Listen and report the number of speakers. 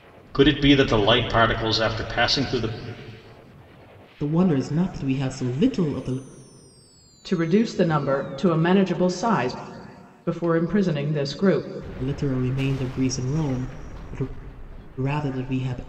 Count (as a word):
three